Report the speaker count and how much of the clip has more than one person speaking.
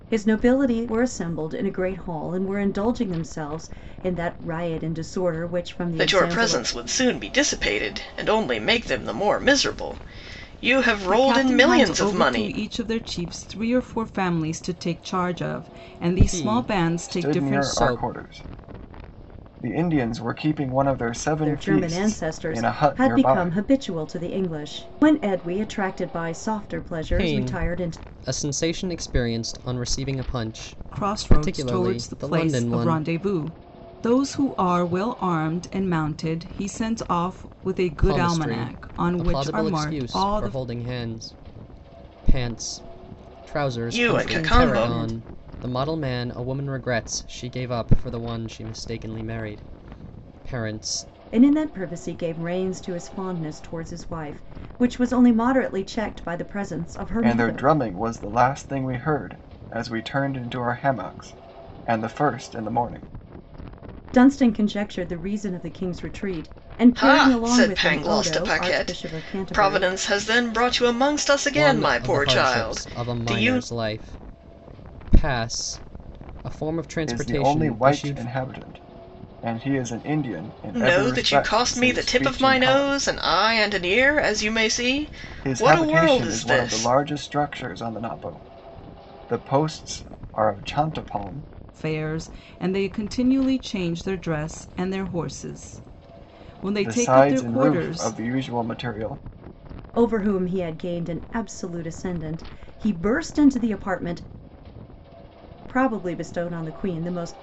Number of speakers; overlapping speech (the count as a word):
five, about 24%